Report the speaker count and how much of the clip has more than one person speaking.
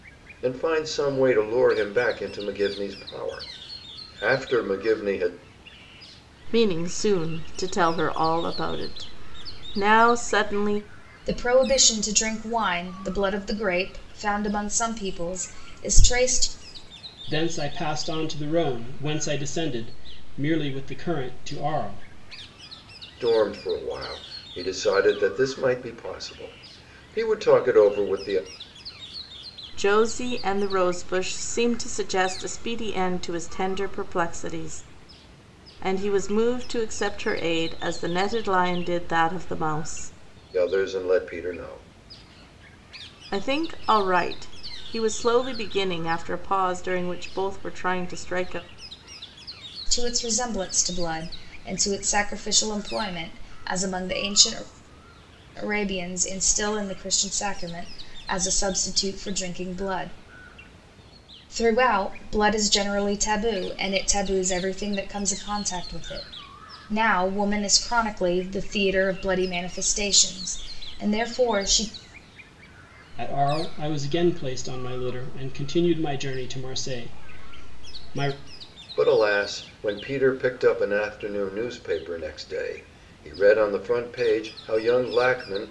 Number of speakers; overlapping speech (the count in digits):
4, no overlap